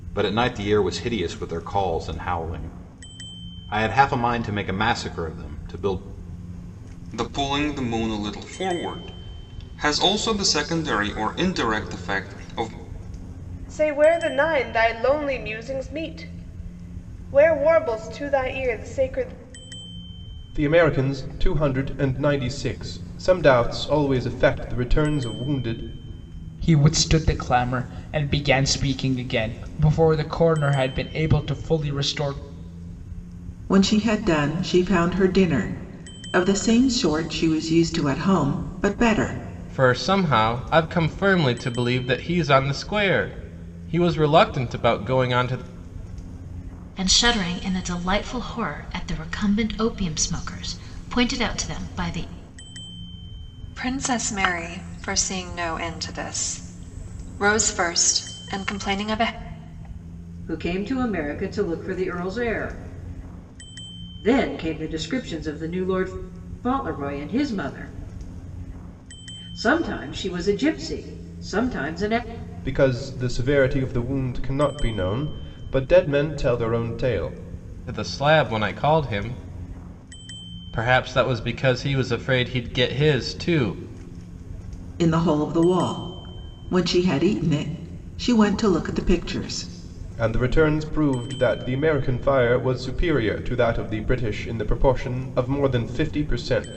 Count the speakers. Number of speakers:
10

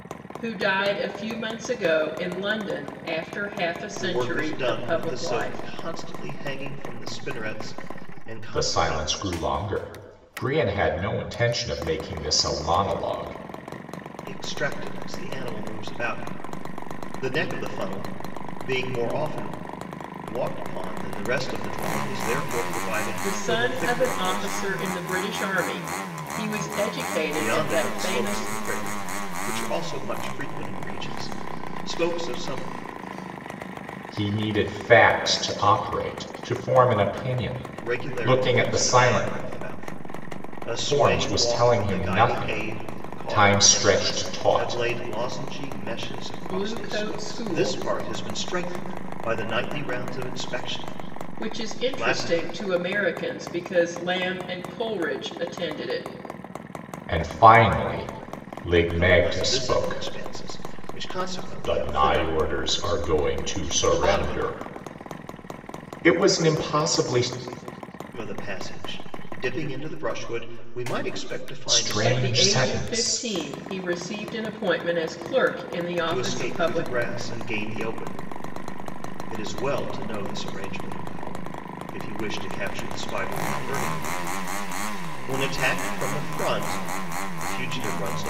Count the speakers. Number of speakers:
3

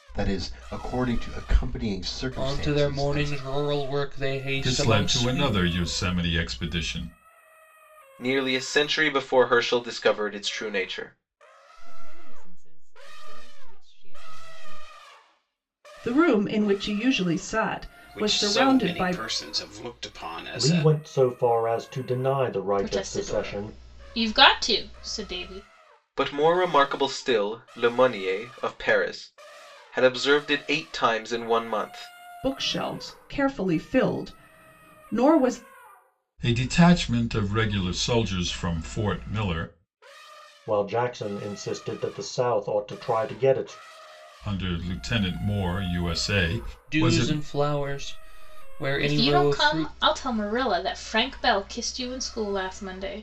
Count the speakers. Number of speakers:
9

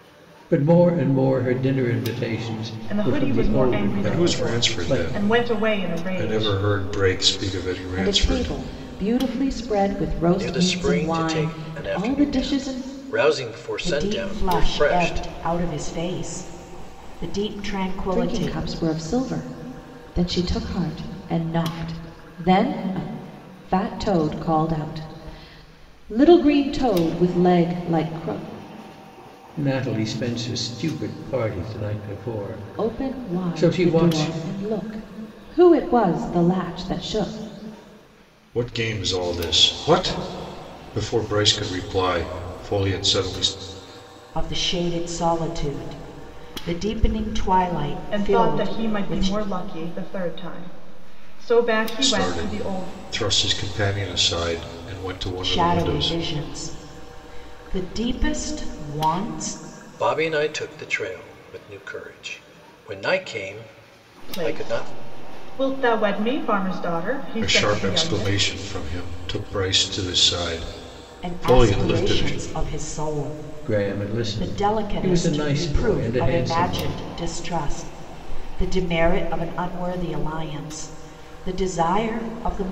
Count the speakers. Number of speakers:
6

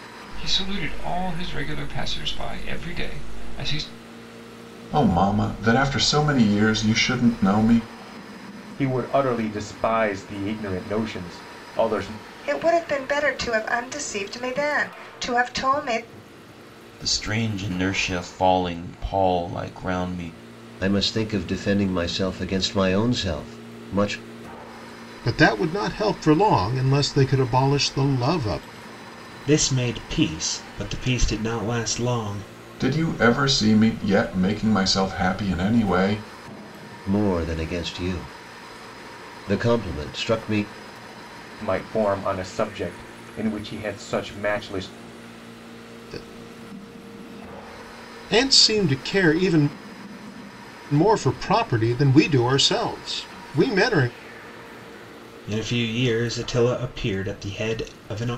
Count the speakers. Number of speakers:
8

